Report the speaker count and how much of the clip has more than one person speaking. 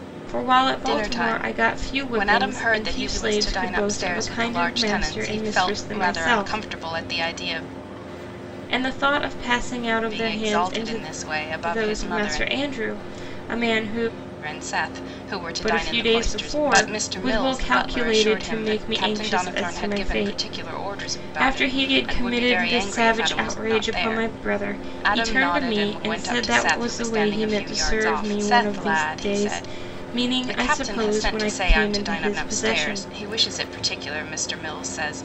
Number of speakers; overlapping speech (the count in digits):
2, about 69%